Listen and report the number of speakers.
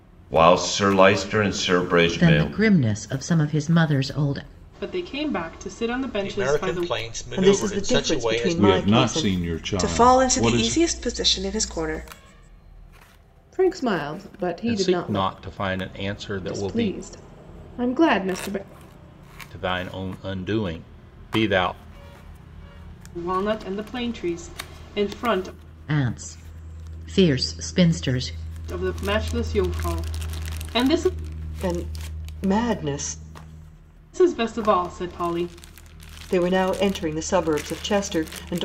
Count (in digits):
9